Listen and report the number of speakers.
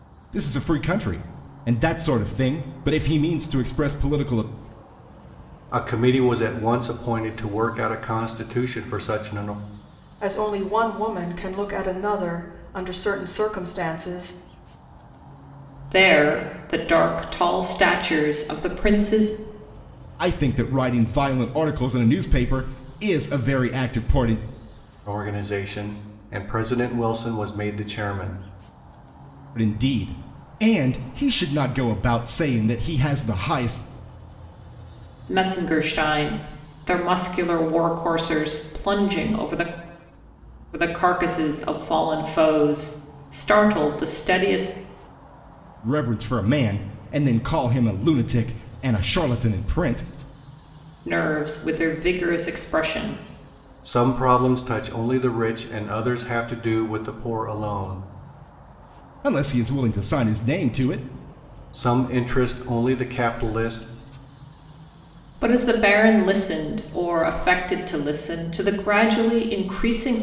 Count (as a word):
four